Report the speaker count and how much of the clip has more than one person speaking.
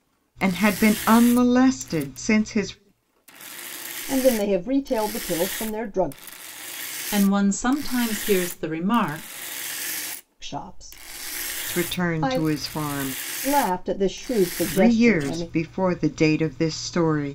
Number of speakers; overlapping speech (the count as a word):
three, about 10%